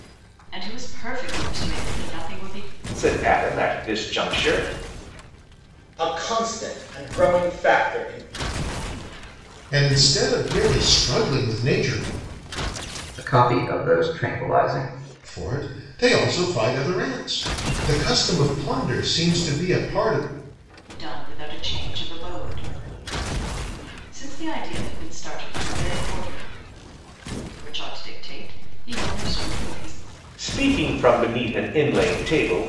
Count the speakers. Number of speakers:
5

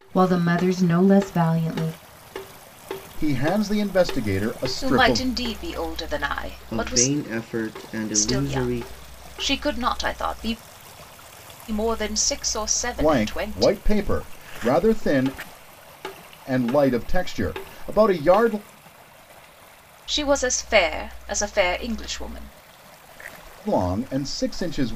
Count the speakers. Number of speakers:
4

